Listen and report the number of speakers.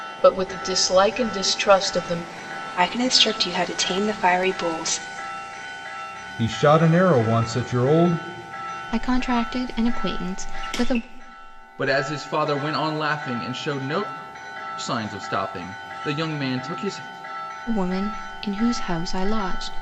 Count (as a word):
five